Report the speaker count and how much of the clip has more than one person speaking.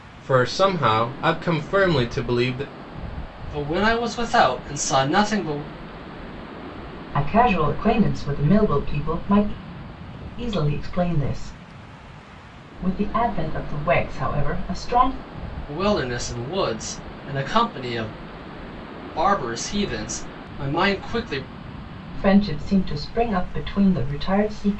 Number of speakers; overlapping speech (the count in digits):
3, no overlap